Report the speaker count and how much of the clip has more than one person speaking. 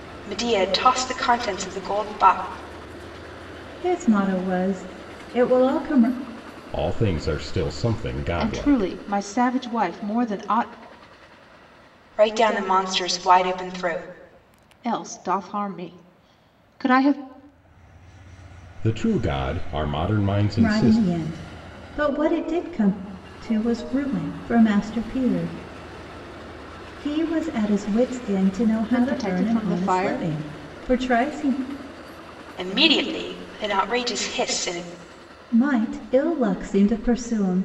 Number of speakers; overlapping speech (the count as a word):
four, about 7%